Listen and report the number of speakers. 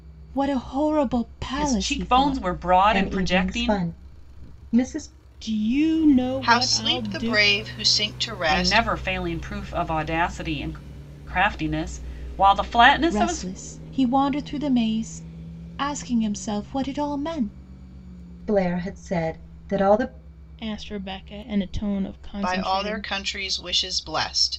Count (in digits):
5